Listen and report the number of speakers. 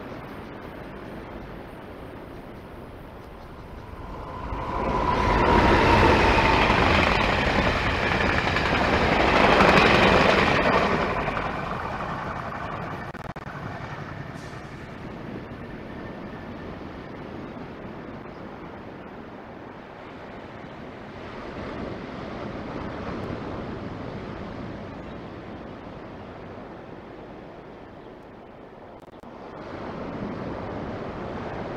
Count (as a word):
zero